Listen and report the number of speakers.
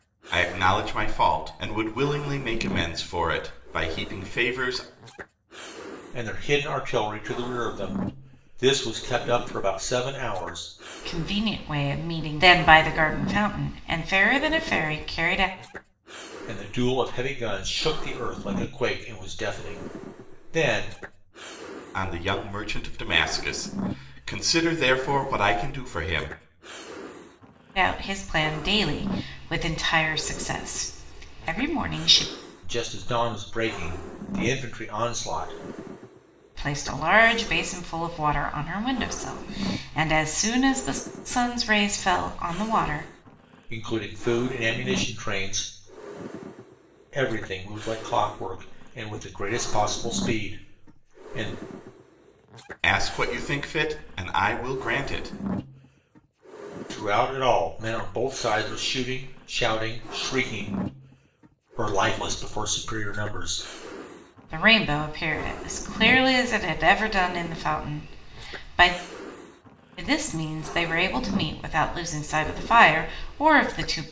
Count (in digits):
3